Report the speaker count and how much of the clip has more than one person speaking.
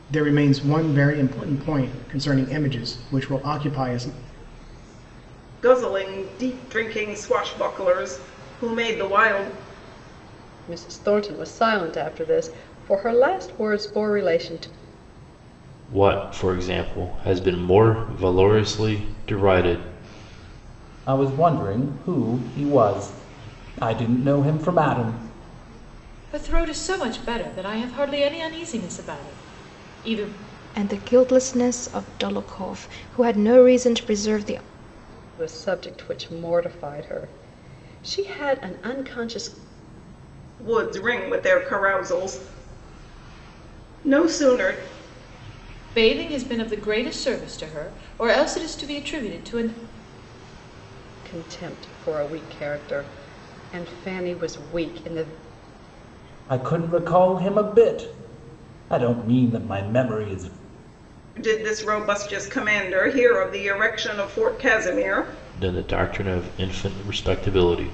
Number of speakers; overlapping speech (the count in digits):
7, no overlap